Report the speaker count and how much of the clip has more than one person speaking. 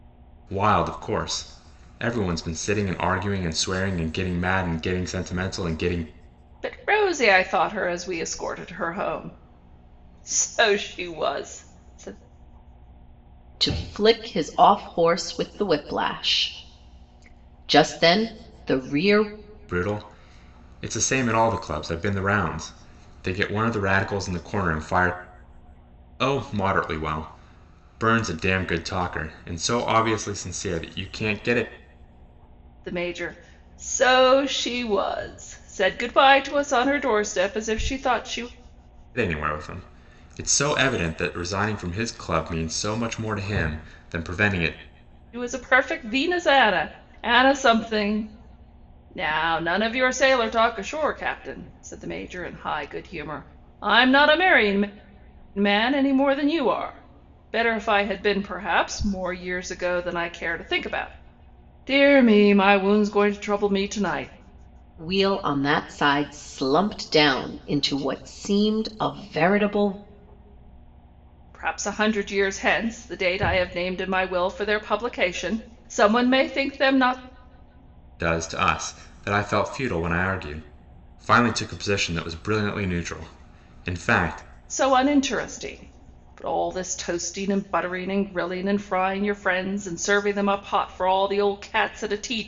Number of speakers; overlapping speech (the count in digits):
3, no overlap